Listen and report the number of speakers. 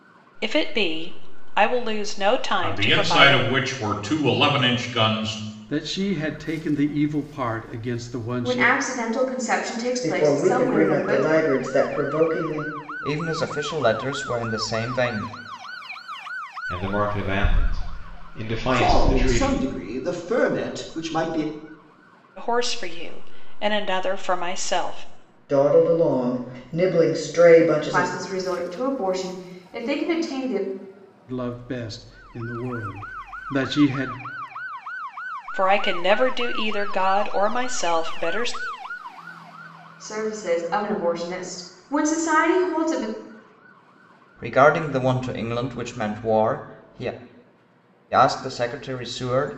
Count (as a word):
eight